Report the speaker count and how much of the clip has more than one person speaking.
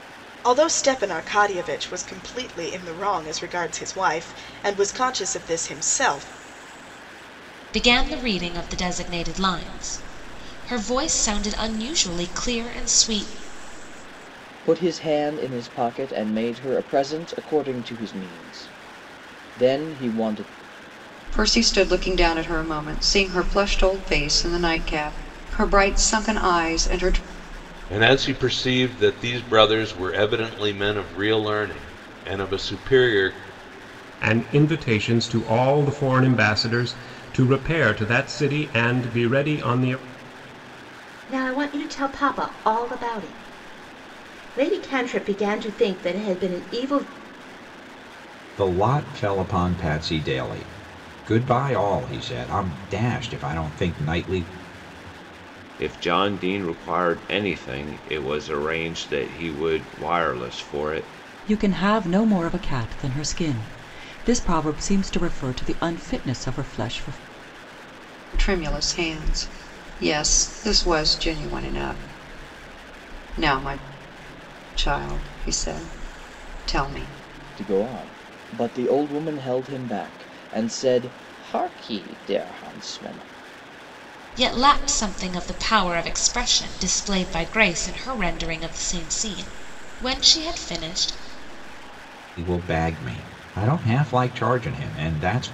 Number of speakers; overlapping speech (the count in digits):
10, no overlap